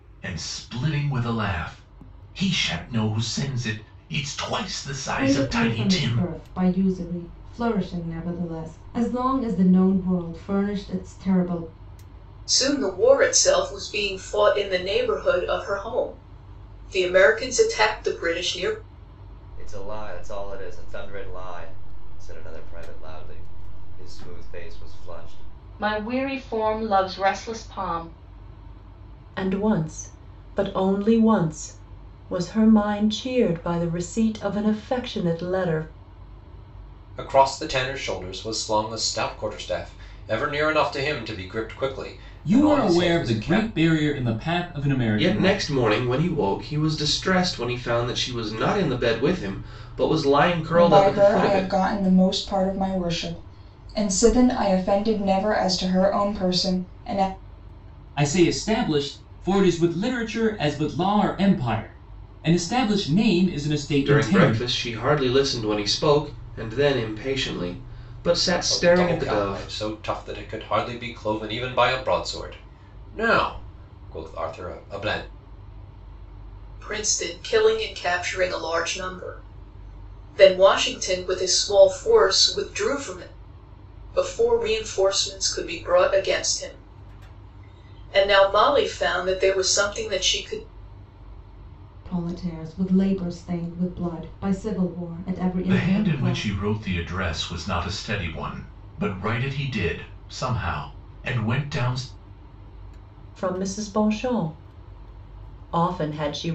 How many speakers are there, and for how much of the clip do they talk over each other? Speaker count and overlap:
ten, about 7%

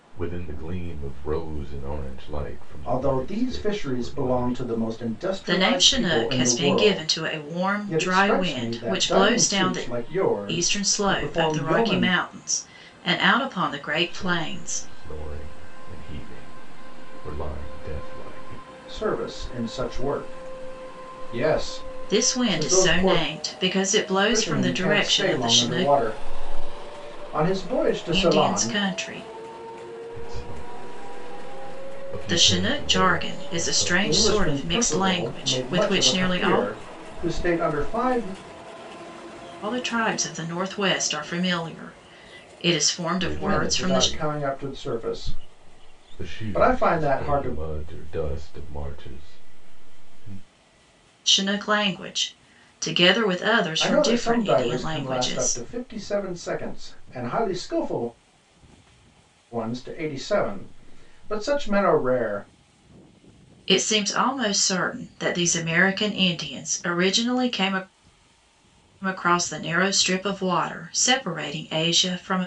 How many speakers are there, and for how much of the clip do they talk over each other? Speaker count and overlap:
three, about 28%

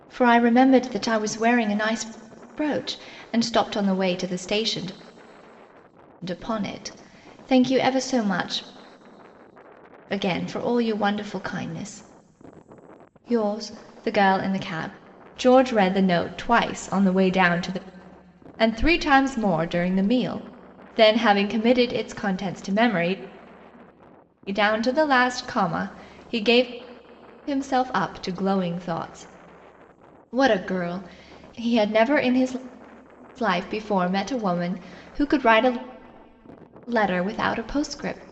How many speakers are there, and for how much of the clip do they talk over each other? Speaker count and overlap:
one, no overlap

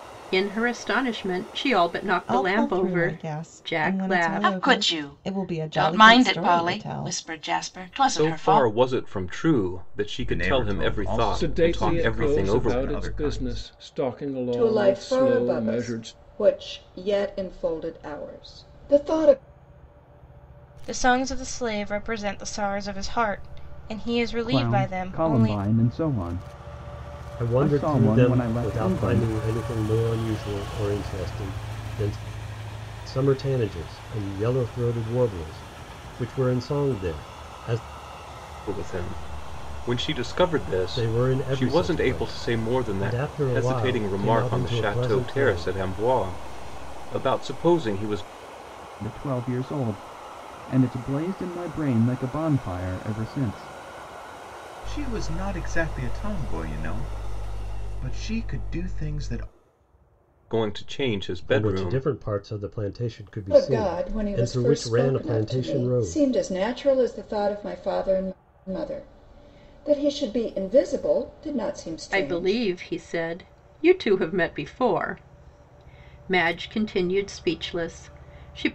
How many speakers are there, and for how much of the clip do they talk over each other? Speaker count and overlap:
ten, about 29%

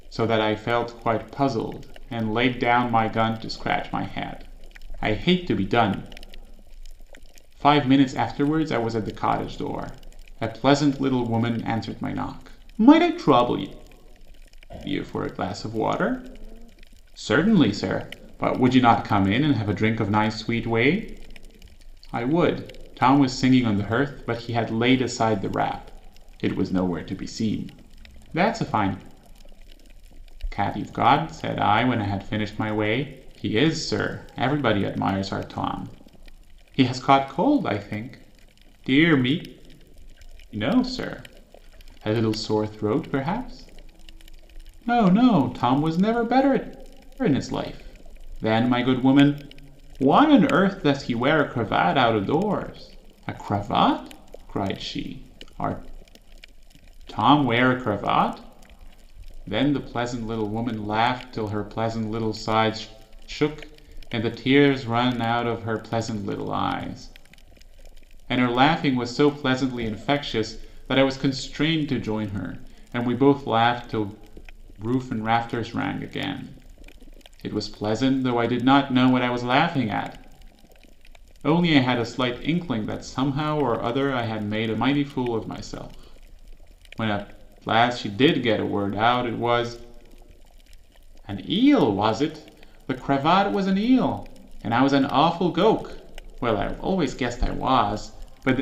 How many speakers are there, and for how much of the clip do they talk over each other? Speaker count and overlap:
one, no overlap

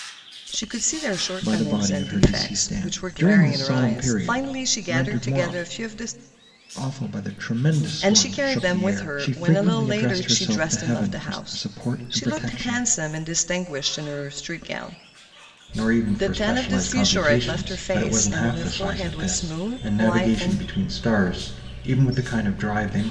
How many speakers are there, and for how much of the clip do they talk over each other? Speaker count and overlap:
two, about 57%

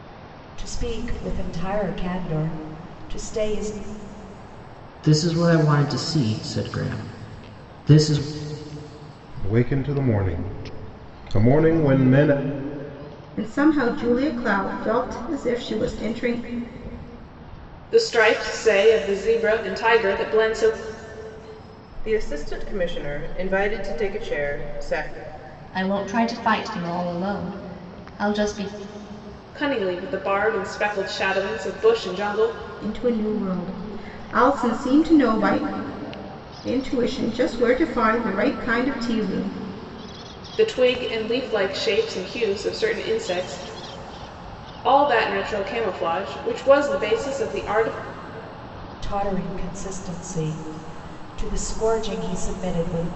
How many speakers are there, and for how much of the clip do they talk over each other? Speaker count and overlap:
seven, no overlap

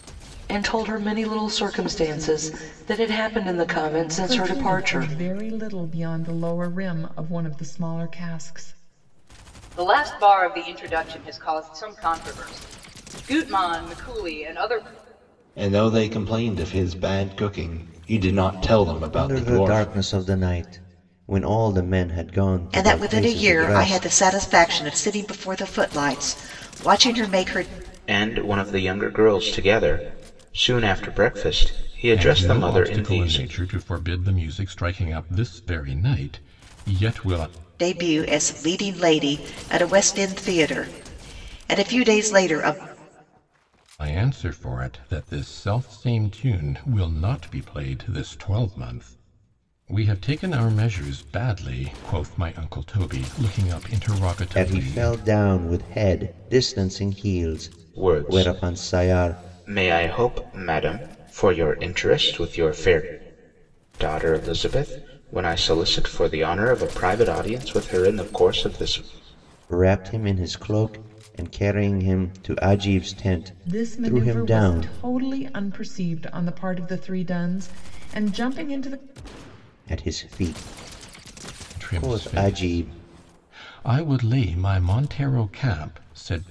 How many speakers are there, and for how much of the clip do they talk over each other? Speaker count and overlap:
eight, about 11%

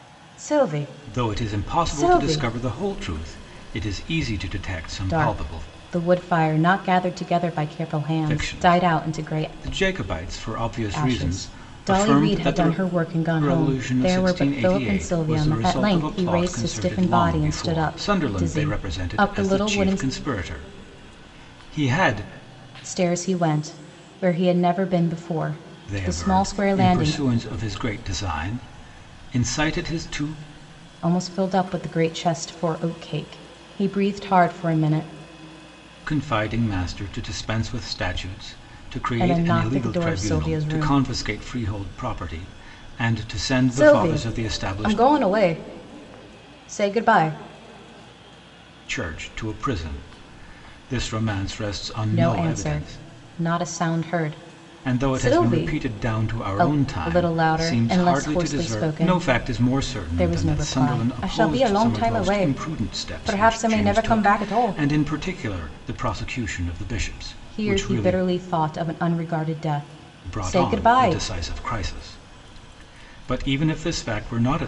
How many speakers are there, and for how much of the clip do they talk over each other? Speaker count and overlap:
two, about 38%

